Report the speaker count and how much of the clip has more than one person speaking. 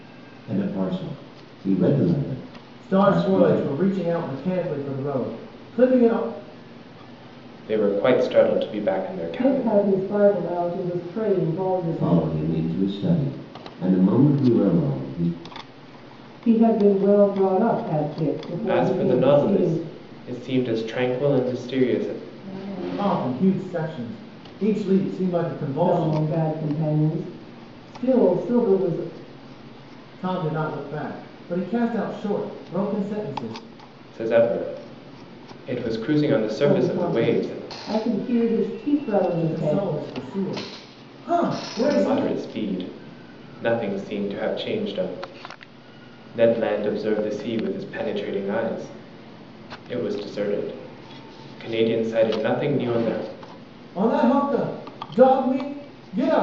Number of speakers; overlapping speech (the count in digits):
4, about 10%